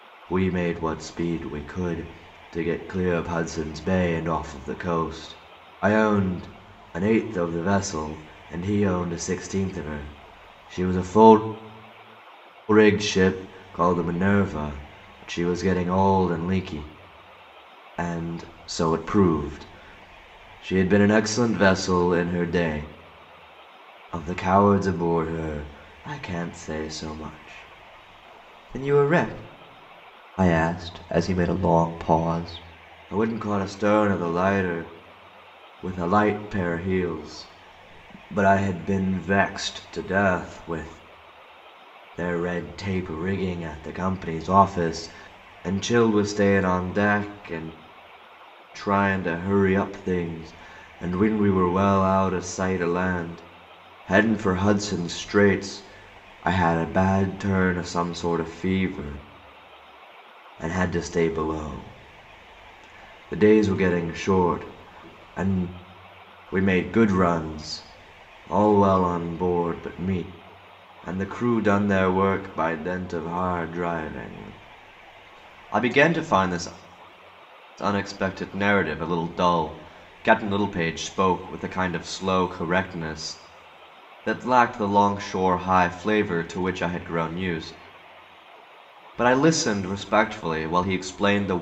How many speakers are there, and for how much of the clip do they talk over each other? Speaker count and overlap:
one, no overlap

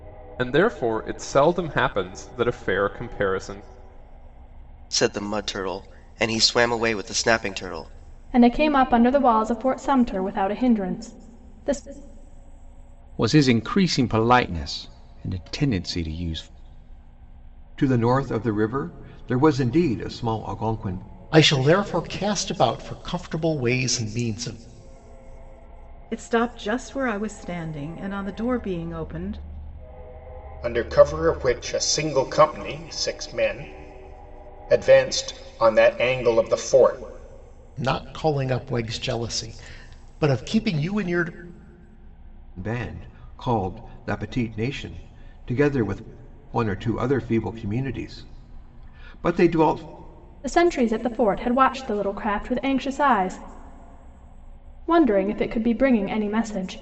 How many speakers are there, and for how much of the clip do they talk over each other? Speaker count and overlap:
eight, no overlap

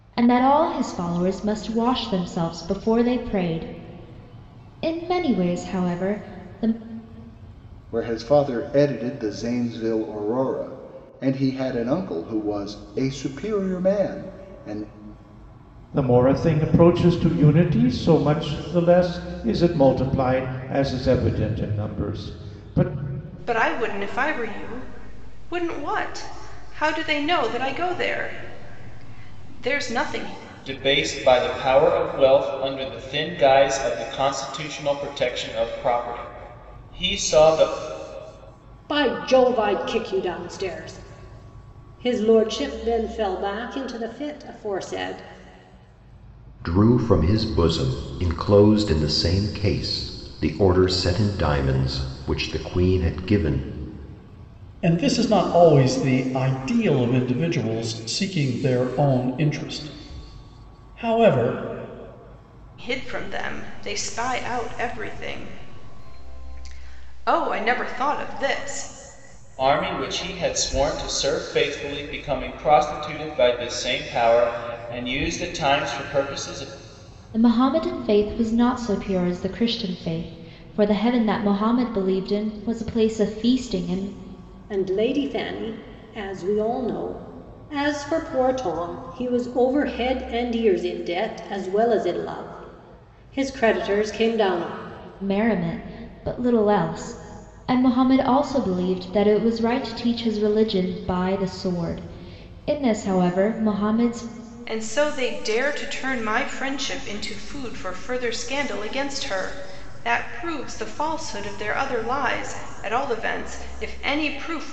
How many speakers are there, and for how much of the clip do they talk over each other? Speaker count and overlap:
eight, no overlap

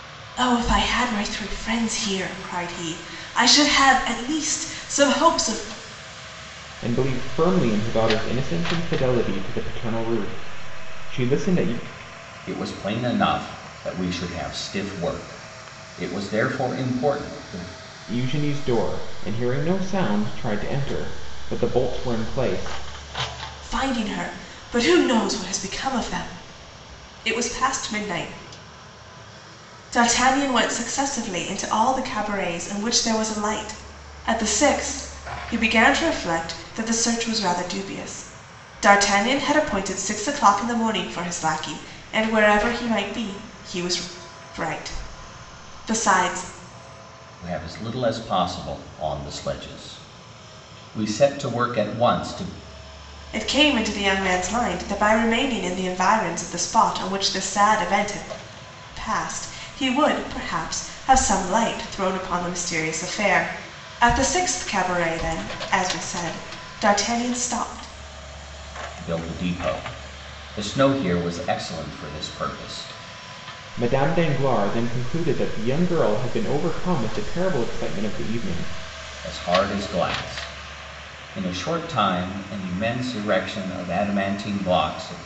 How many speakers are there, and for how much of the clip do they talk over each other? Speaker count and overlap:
three, no overlap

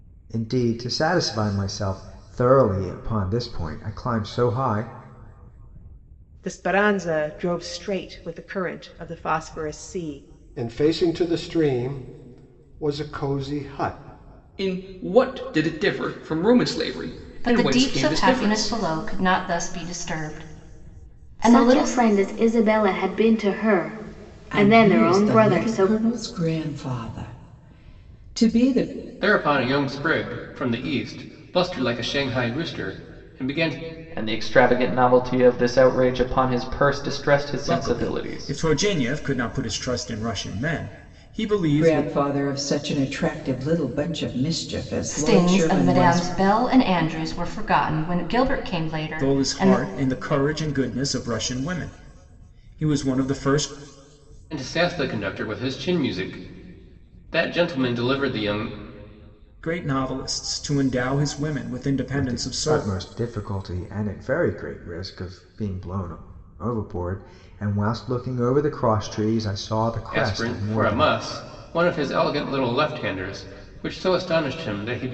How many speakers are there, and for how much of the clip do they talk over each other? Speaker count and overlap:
ten, about 11%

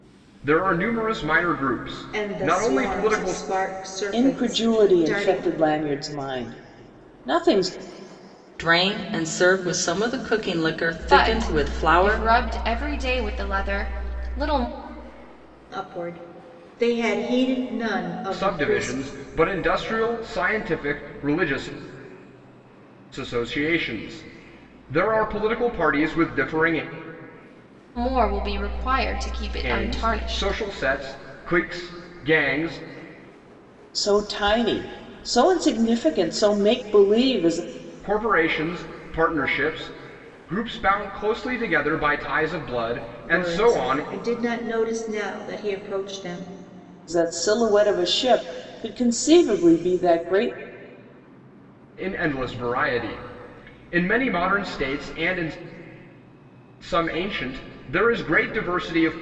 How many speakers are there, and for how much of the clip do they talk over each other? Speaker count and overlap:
five, about 11%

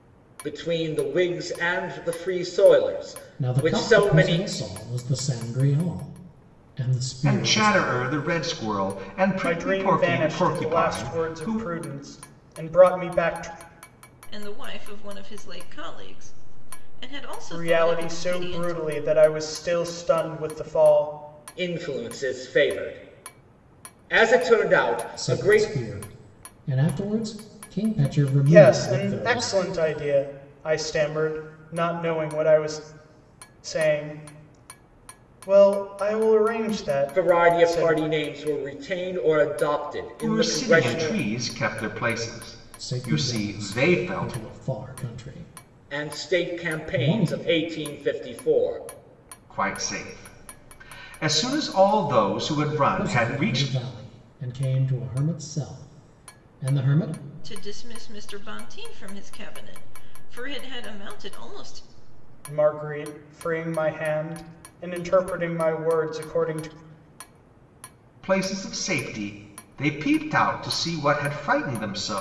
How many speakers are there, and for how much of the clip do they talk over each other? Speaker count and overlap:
five, about 17%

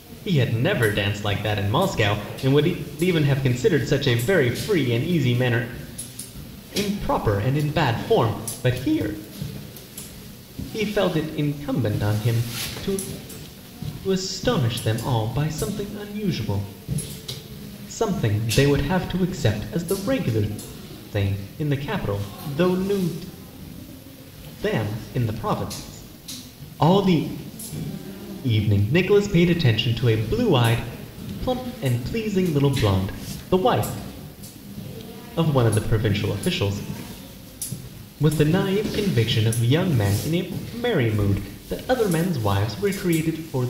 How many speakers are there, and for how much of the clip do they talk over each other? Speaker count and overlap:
one, no overlap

